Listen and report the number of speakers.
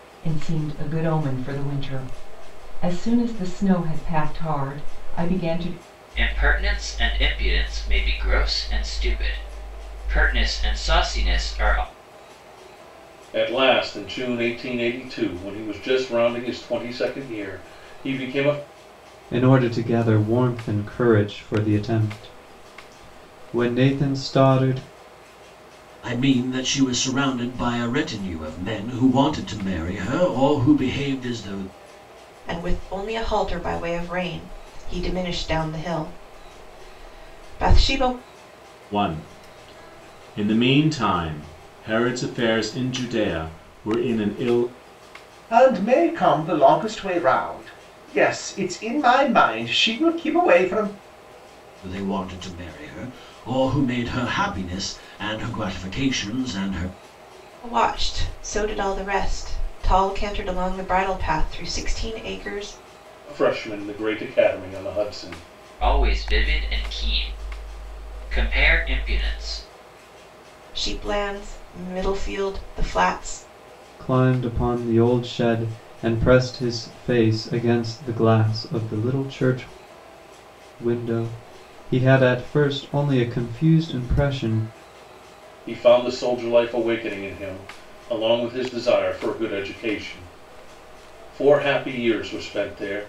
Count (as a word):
eight